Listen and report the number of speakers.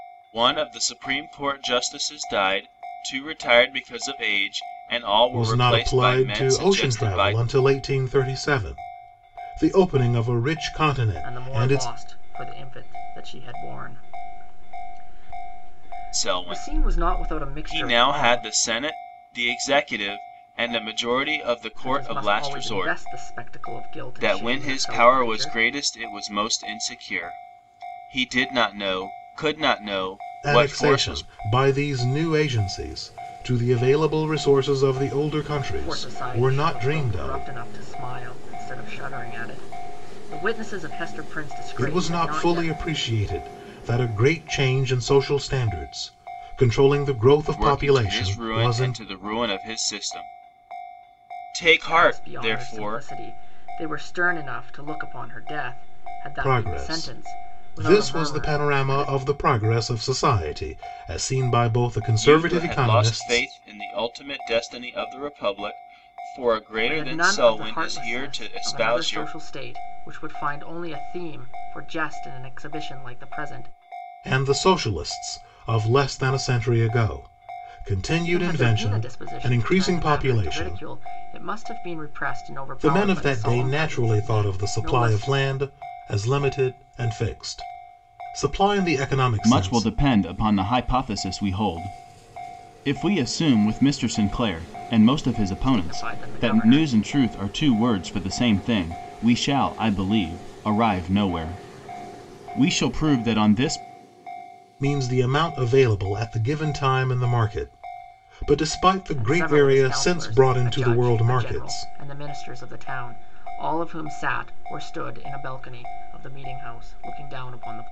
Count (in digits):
3